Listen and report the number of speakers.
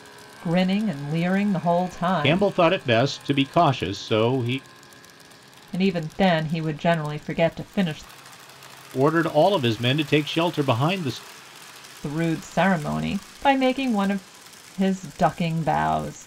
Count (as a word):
two